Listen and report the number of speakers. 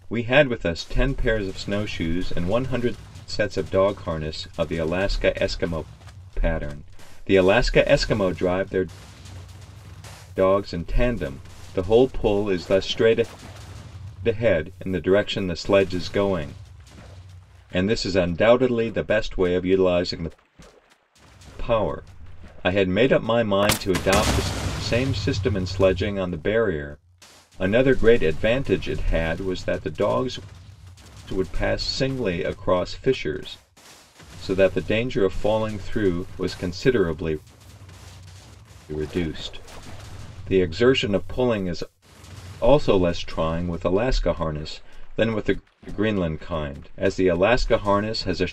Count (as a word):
one